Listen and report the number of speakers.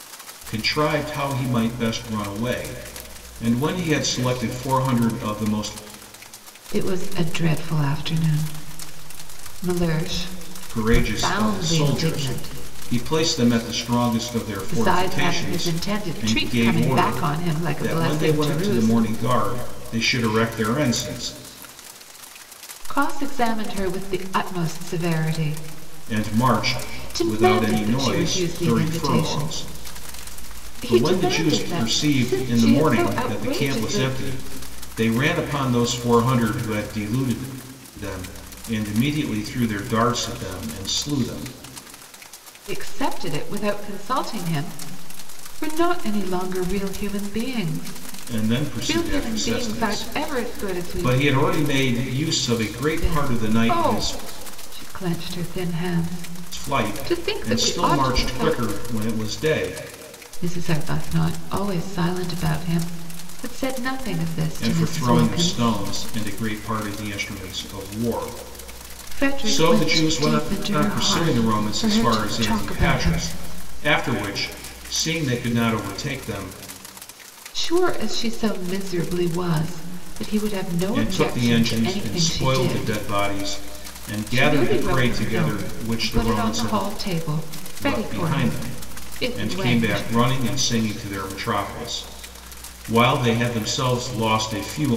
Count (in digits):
2